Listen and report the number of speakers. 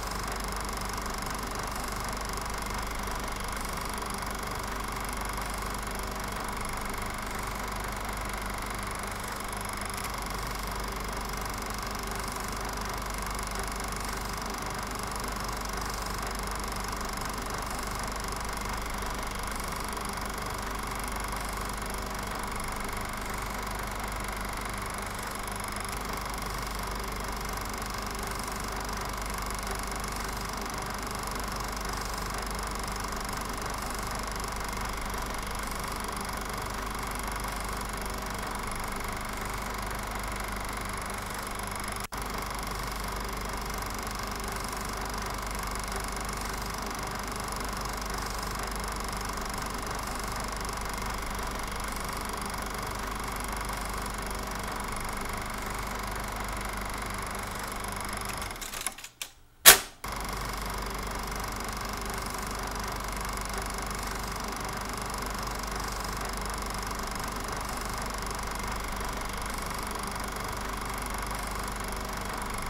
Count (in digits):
0